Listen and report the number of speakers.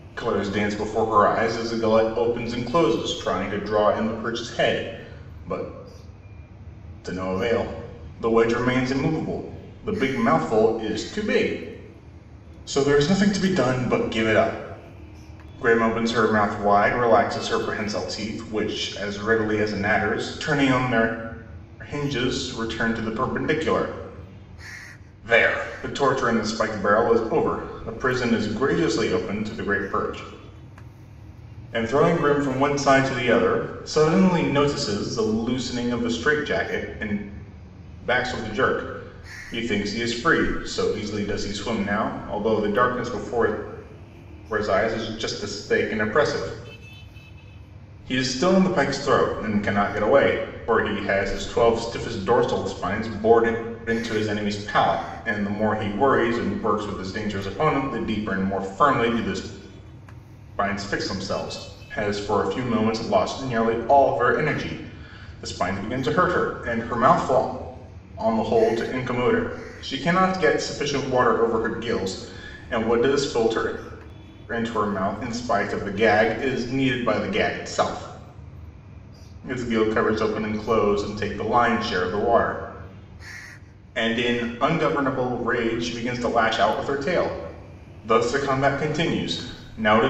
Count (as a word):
one